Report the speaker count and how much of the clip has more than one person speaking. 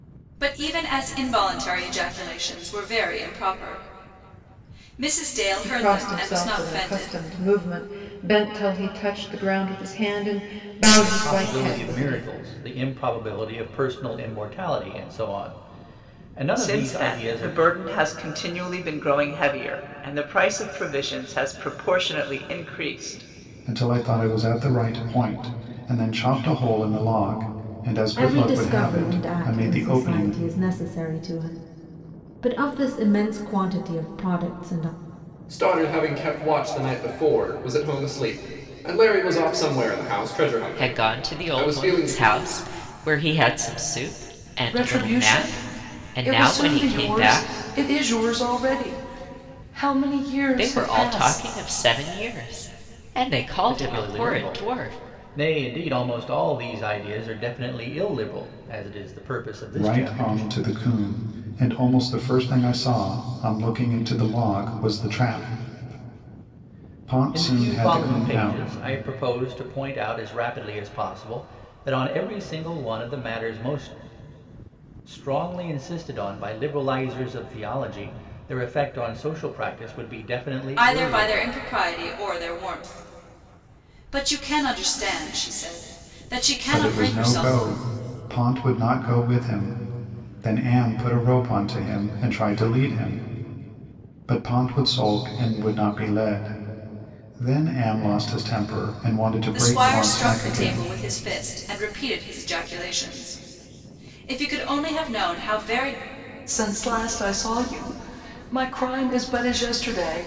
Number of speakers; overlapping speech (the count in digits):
9, about 17%